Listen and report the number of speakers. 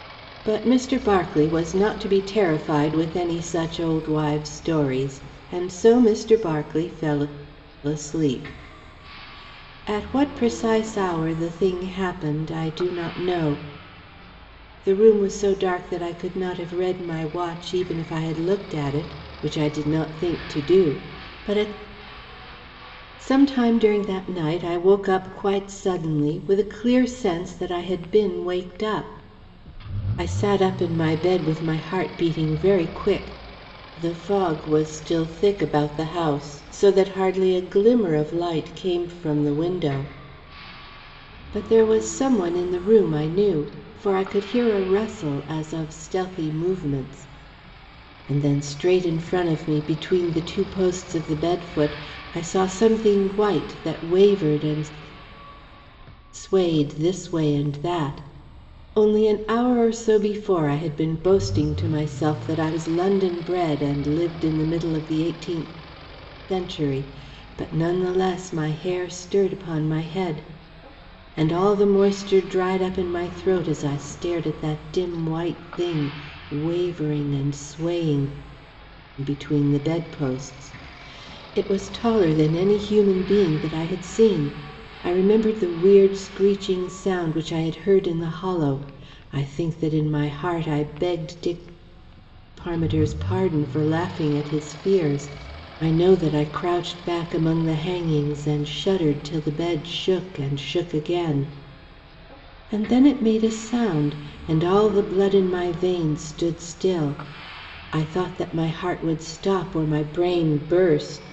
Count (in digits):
1